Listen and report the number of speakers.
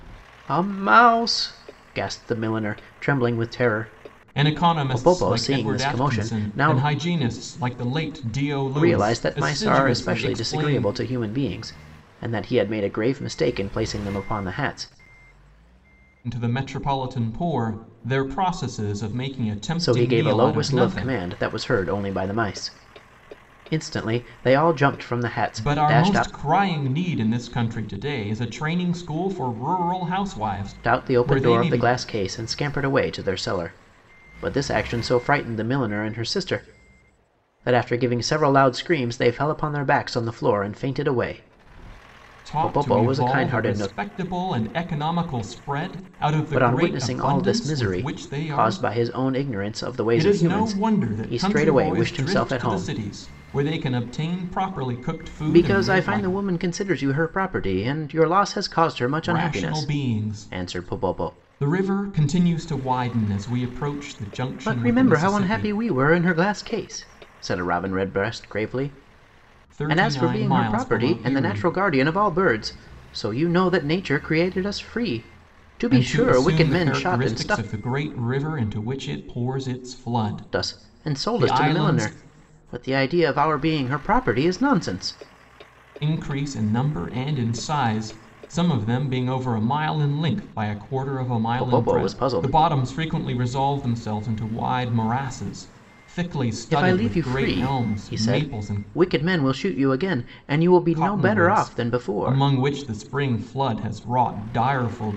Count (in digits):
2